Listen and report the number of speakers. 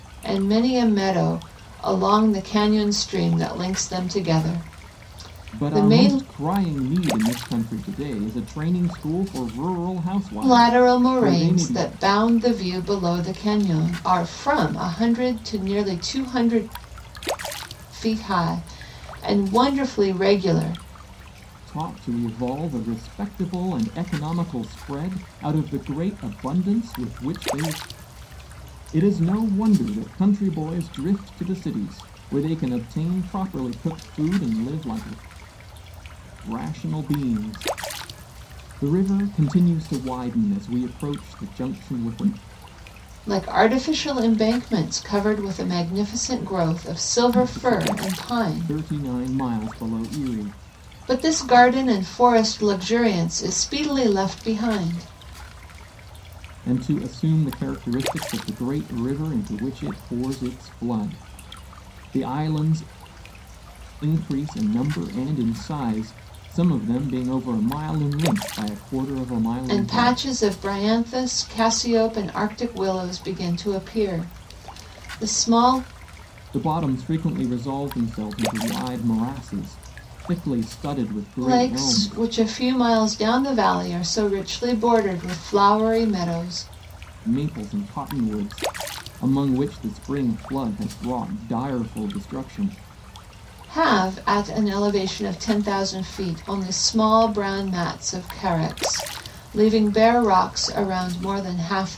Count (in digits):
2